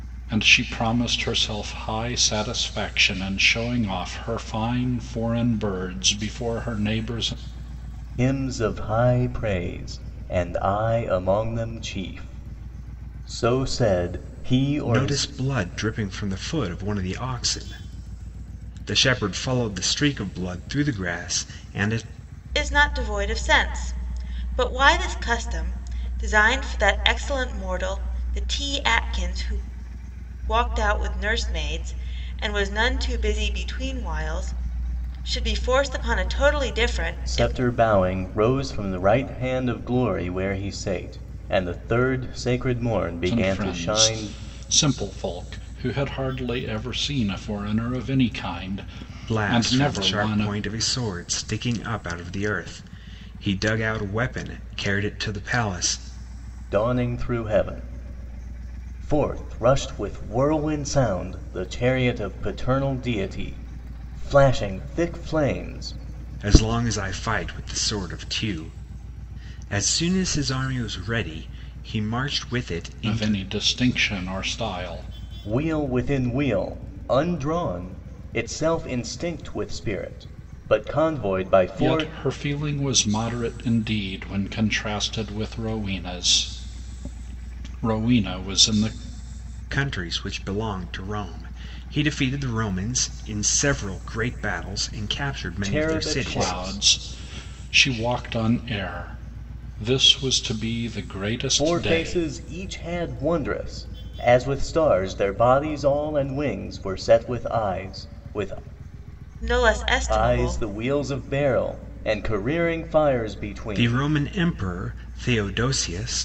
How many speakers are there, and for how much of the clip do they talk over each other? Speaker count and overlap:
4, about 6%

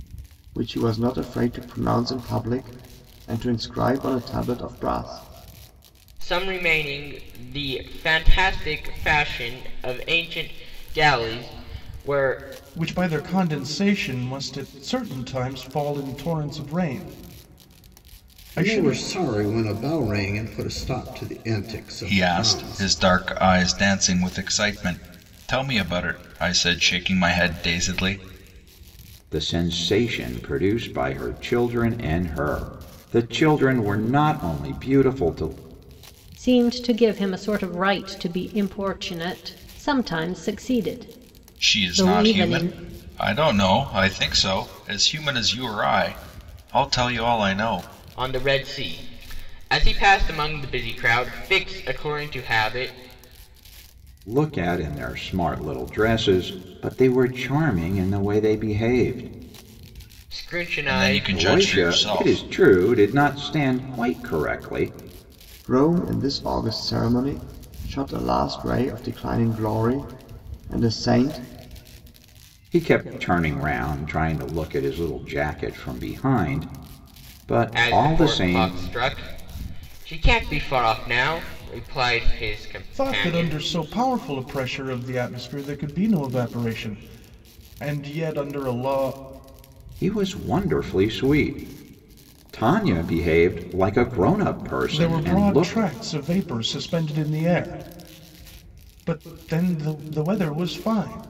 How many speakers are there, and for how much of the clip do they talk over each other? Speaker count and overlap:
7, about 7%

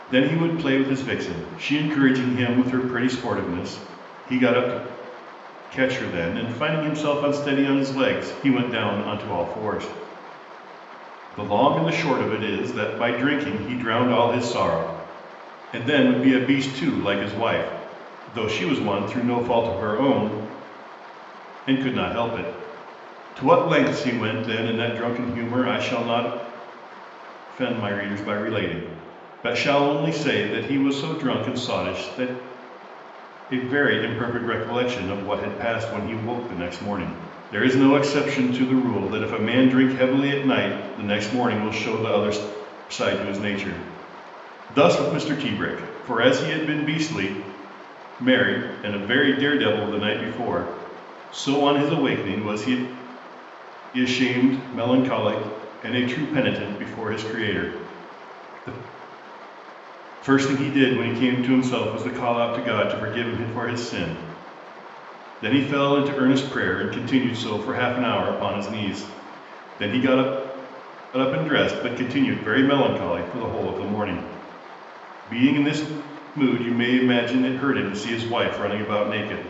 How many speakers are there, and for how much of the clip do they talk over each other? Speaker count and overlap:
1, no overlap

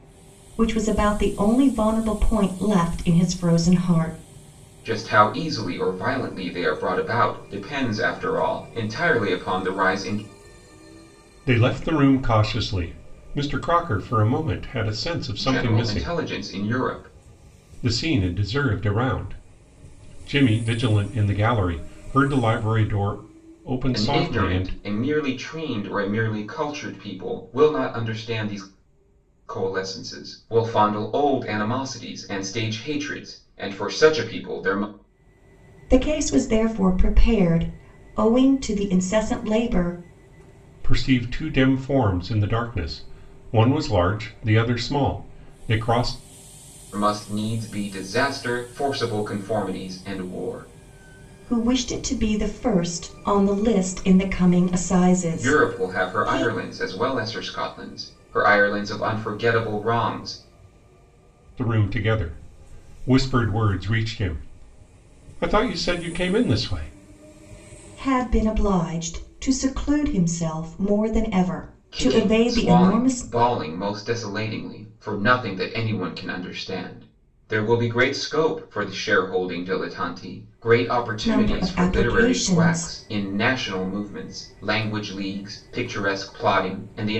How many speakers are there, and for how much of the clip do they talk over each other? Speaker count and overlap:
3, about 7%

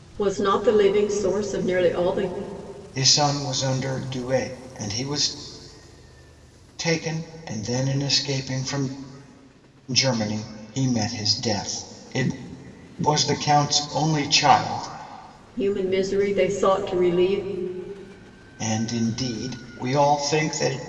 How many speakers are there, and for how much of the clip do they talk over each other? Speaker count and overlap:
2, no overlap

